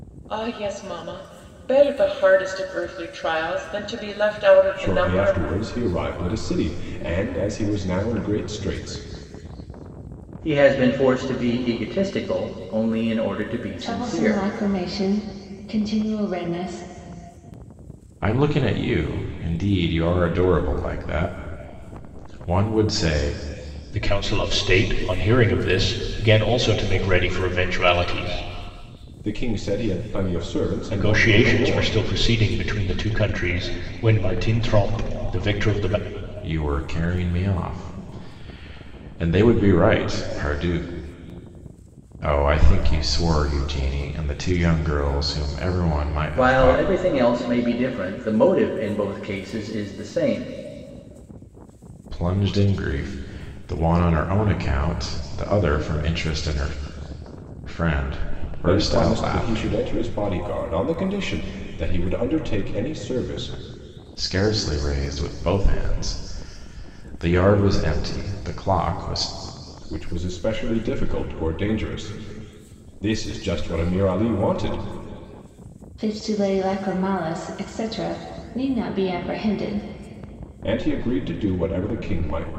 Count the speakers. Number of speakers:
six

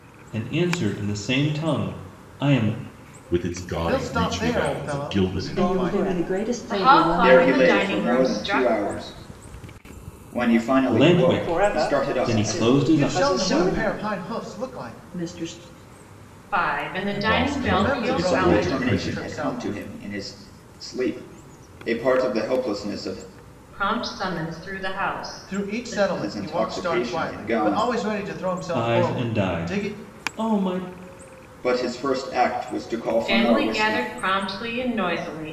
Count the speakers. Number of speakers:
seven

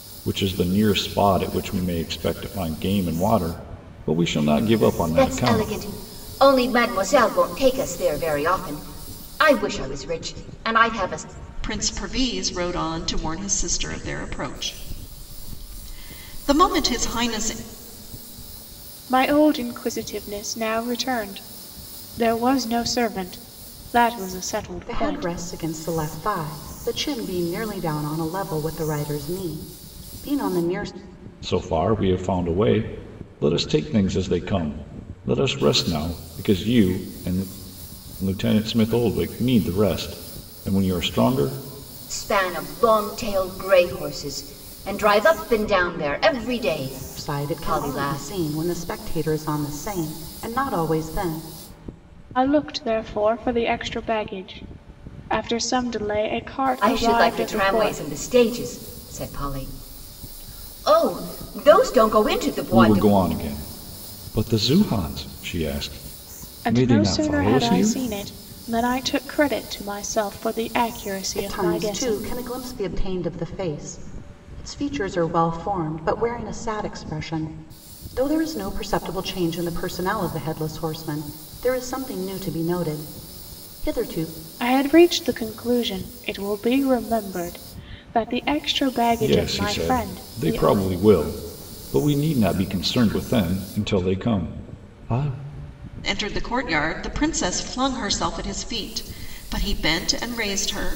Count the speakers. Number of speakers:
five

